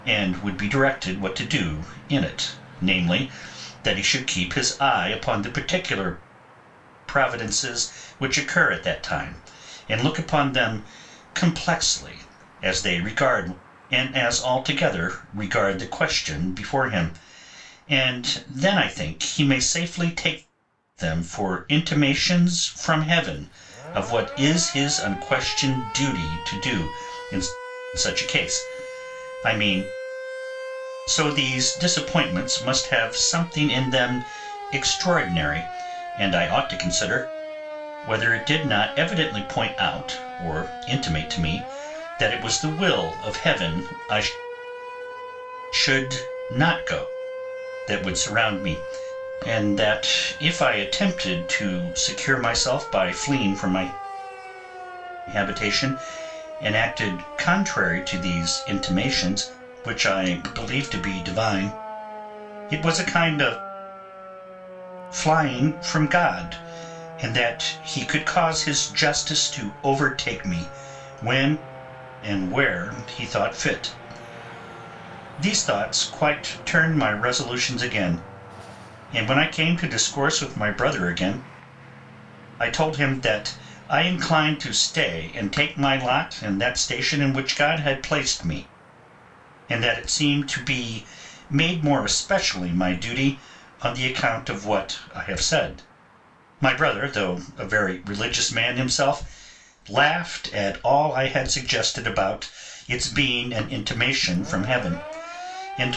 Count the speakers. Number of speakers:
1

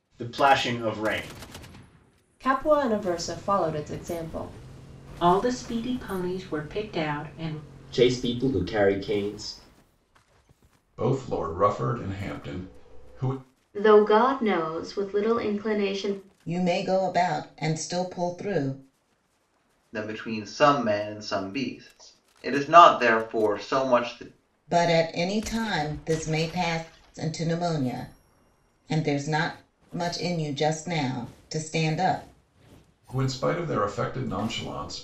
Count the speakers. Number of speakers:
8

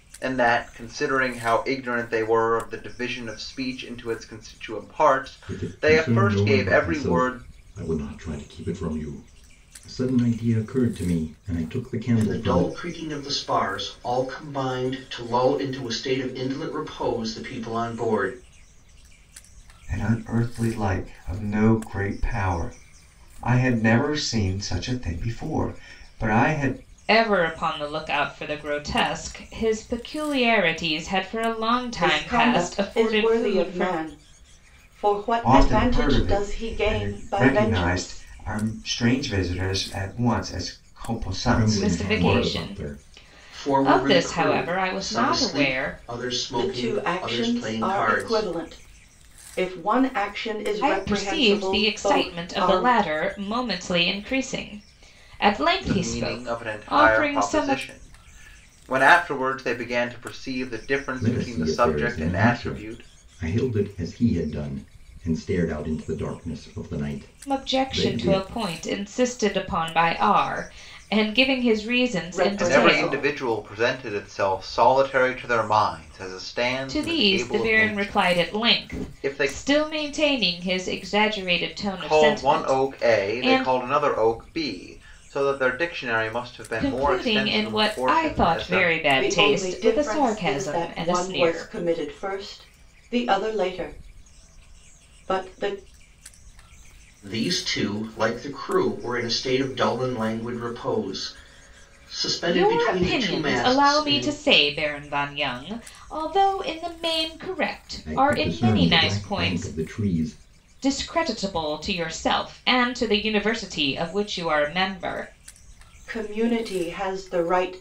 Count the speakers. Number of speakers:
6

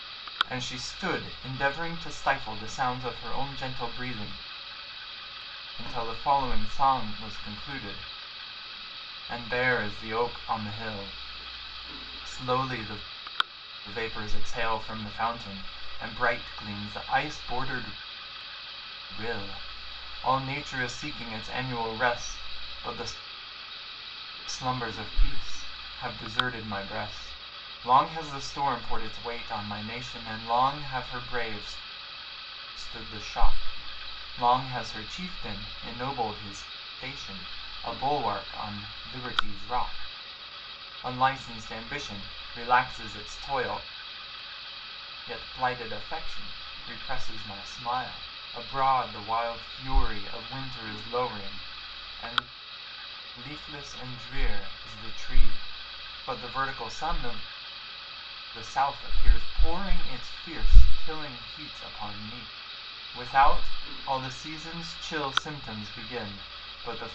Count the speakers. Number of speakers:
1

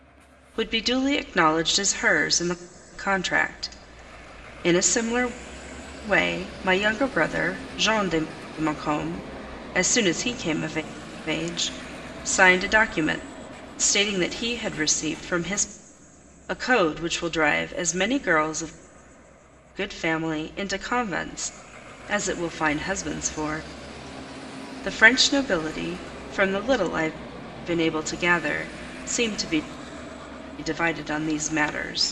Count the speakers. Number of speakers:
1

